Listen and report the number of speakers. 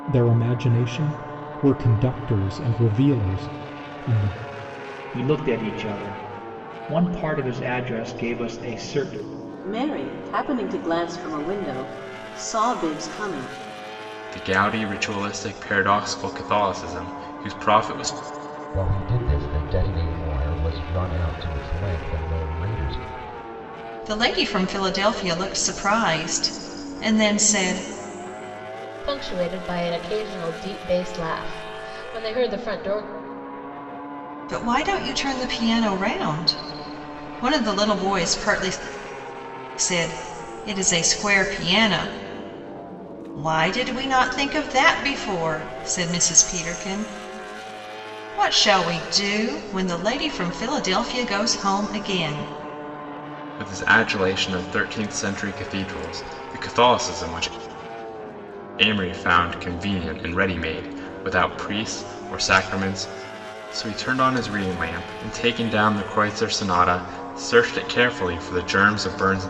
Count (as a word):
seven